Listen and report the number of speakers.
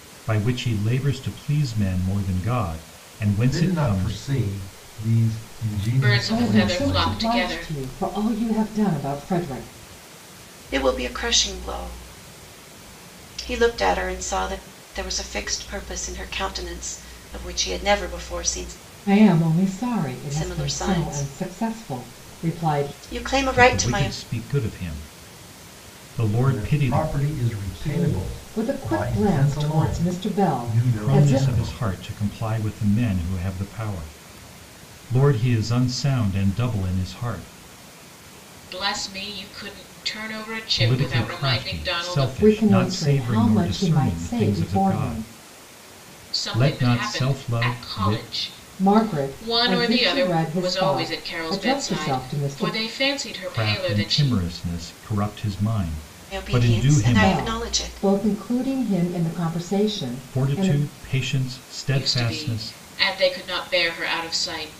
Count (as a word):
five